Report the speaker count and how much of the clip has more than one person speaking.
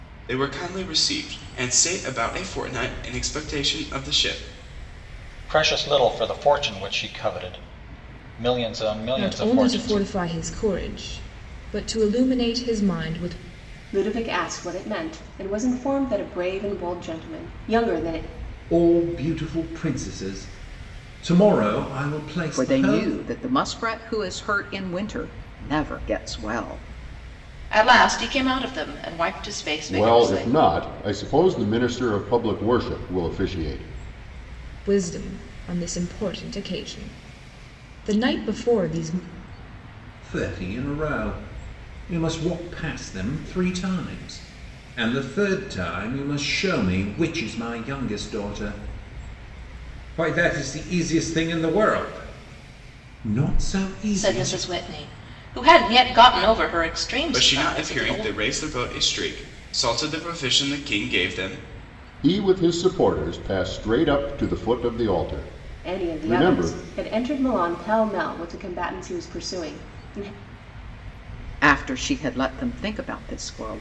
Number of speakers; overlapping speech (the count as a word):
eight, about 6%